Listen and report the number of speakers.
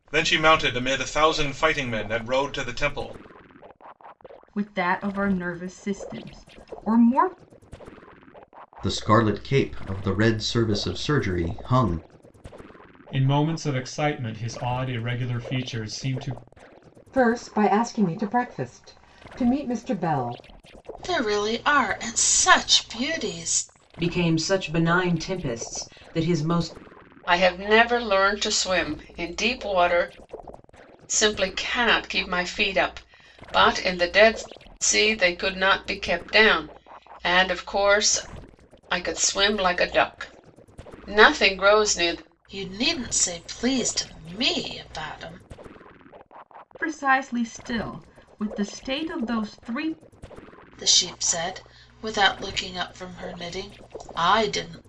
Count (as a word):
eight